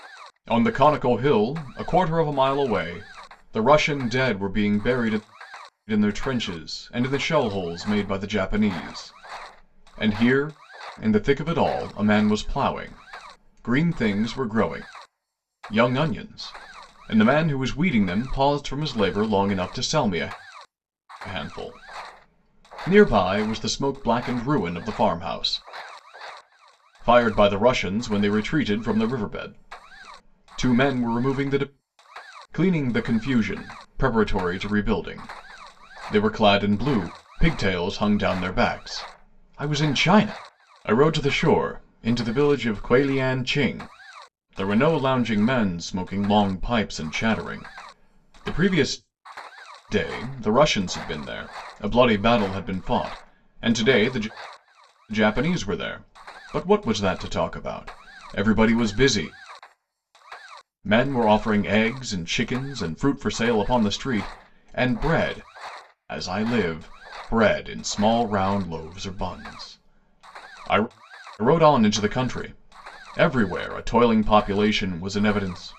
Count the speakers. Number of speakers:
1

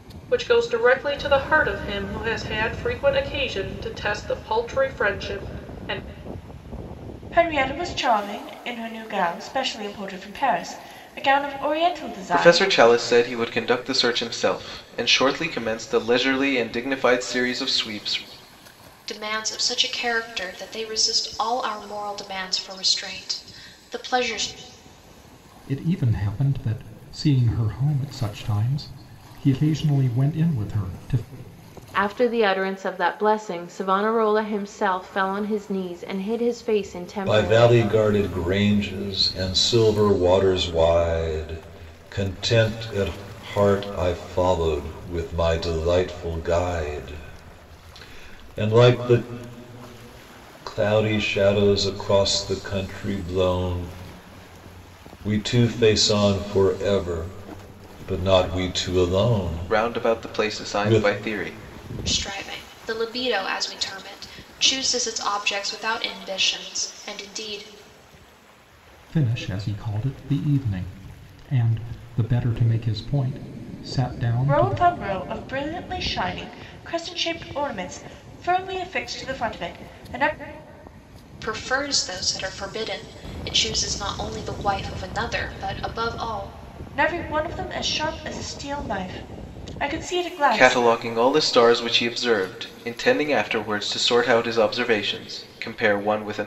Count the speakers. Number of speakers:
7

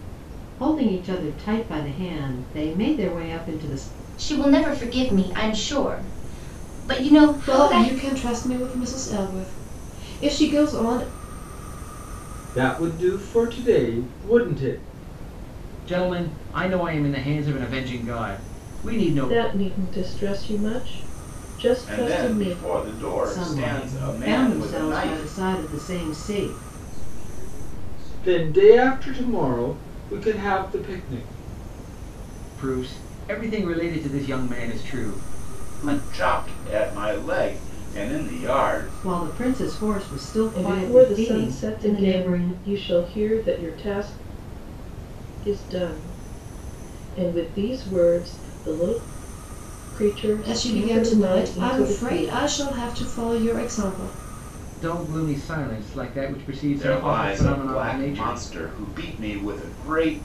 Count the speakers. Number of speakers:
8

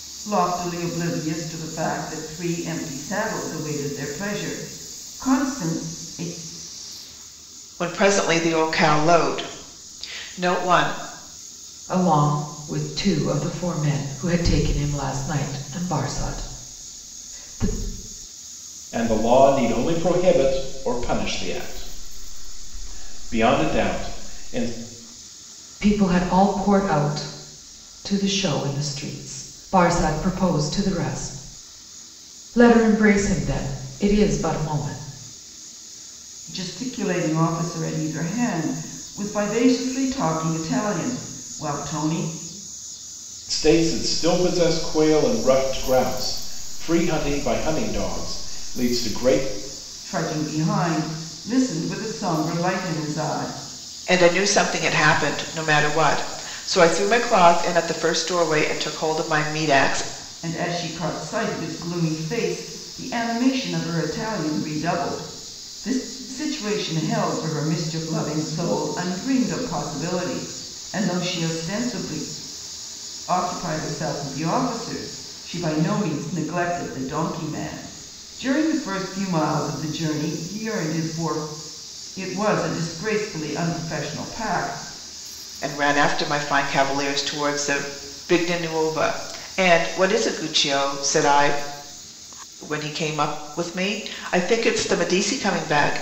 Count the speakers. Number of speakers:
4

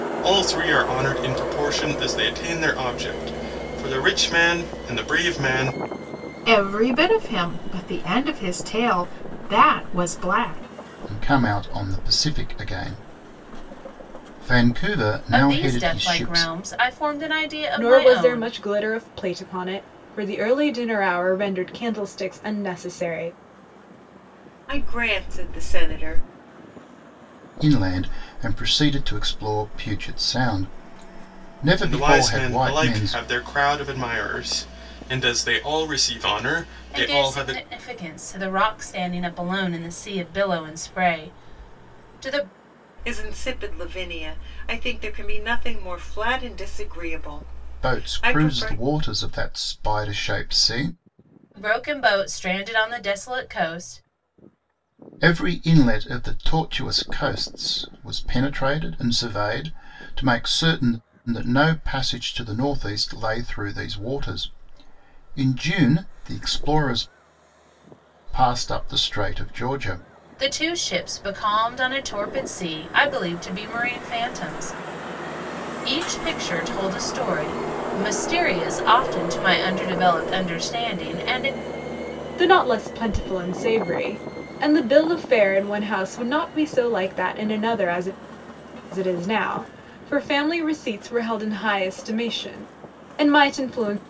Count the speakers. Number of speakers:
6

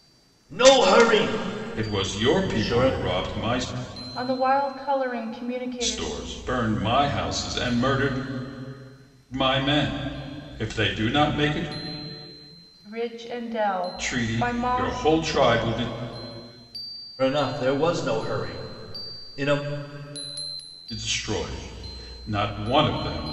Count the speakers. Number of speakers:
3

